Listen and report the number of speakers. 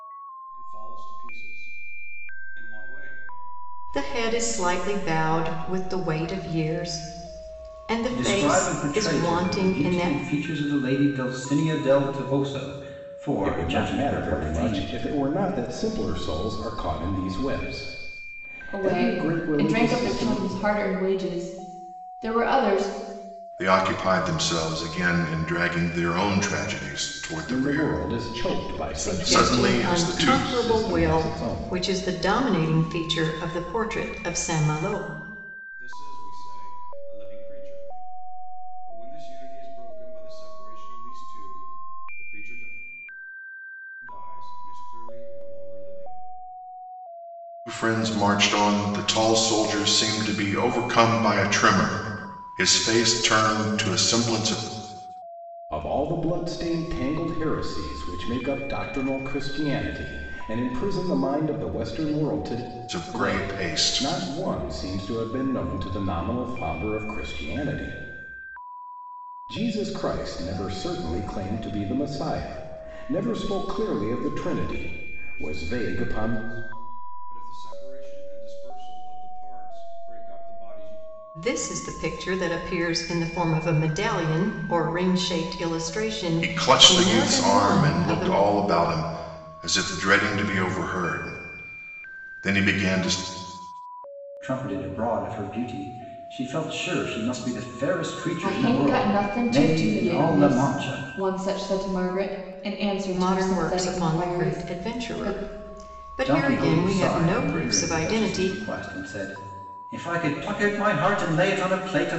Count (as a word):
six